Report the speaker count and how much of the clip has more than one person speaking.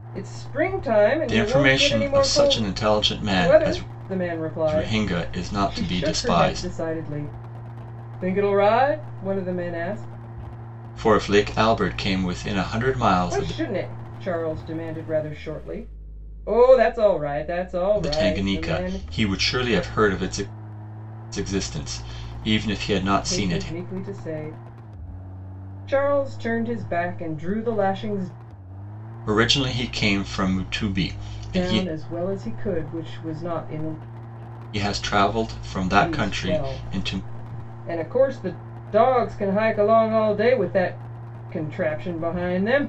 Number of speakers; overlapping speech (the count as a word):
two, about 18%